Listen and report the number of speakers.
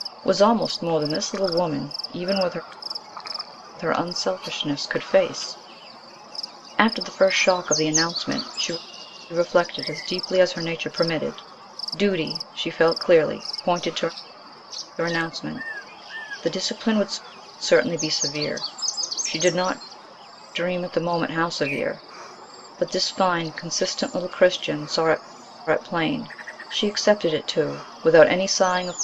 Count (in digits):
1